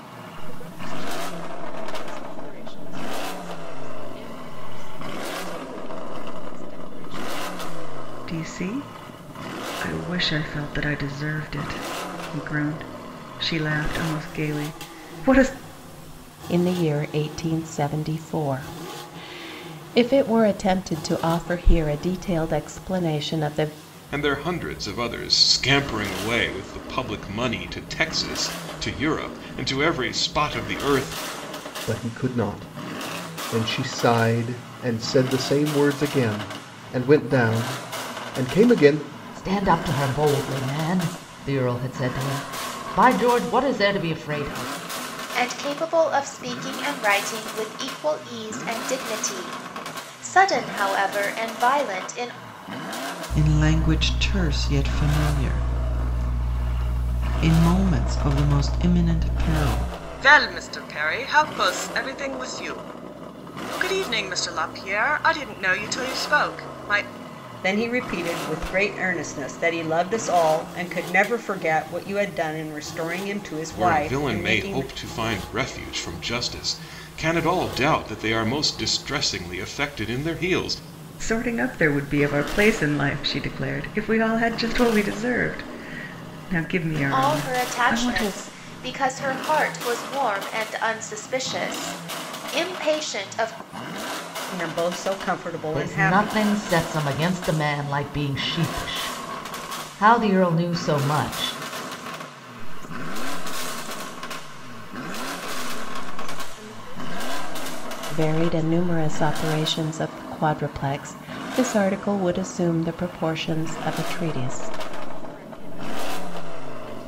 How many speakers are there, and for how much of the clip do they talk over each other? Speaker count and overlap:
10, about 5%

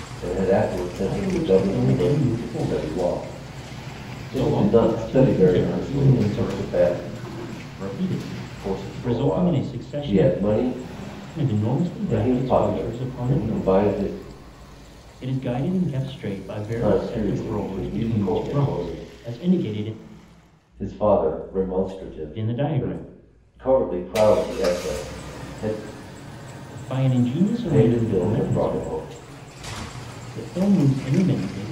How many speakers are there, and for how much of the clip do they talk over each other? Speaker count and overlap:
2, about 38%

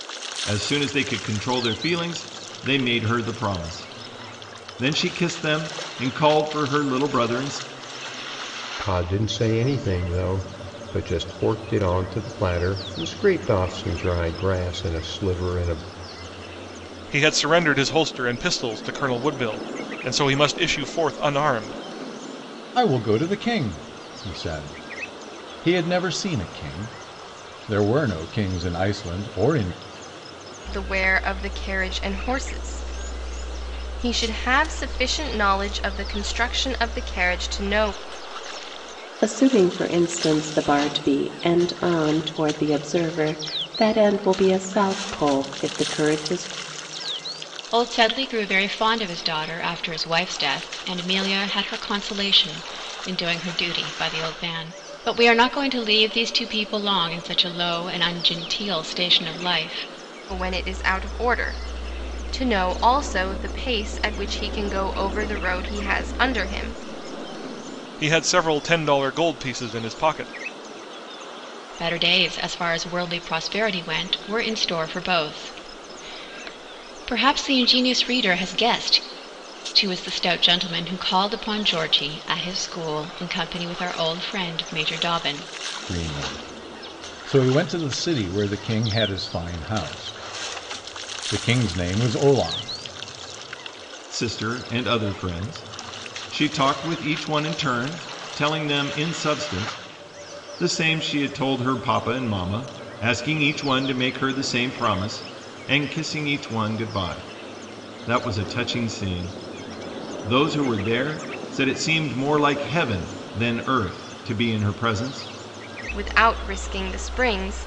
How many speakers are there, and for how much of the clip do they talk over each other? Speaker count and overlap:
7, no overlap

